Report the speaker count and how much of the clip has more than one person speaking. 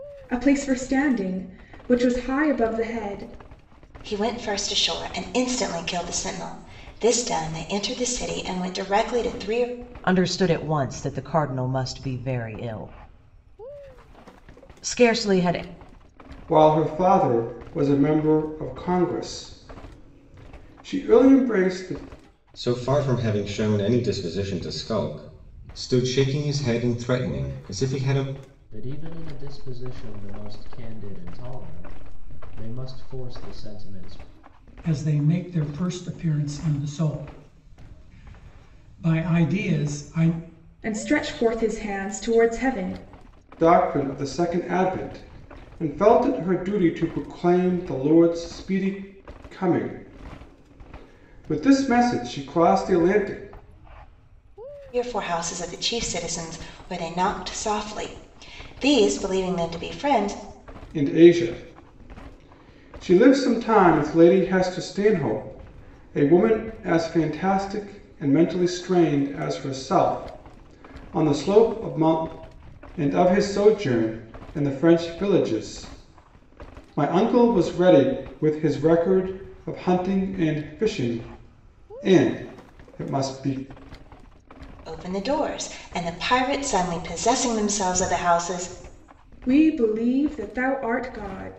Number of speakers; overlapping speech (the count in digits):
7, no overlap